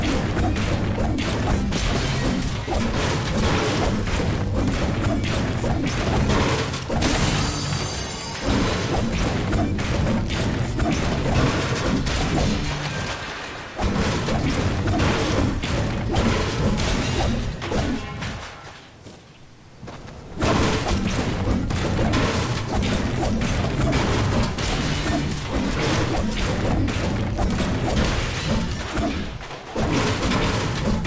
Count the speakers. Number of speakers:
zero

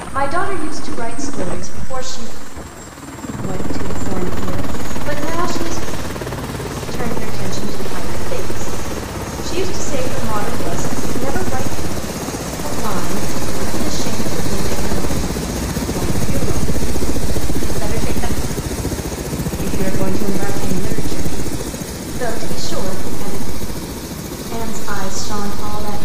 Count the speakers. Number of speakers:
one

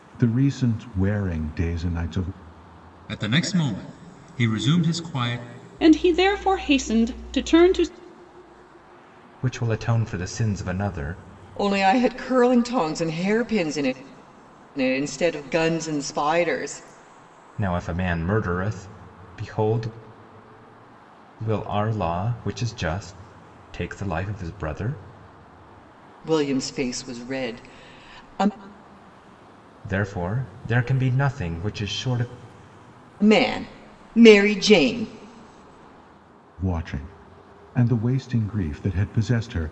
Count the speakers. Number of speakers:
five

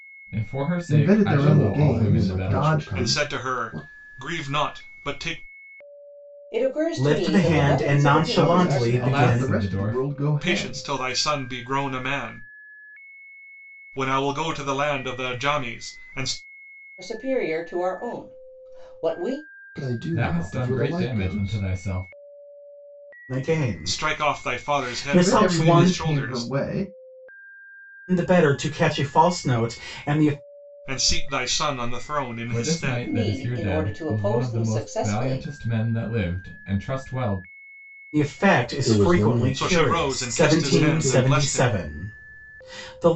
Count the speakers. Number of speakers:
six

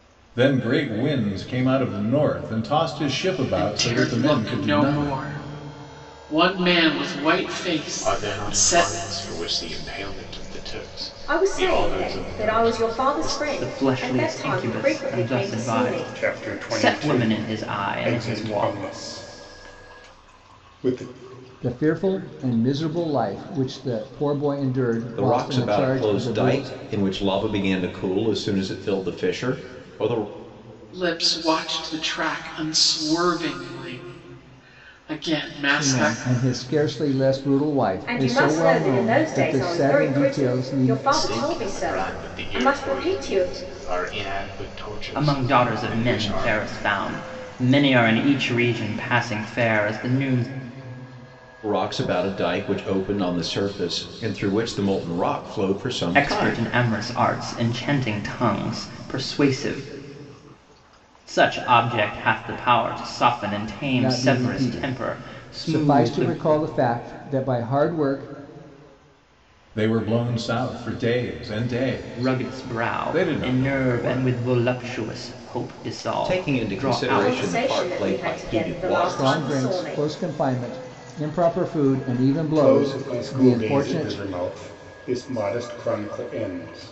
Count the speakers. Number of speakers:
eight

